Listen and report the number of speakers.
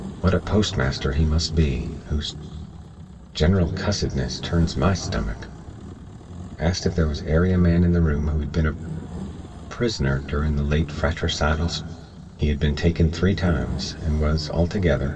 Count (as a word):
one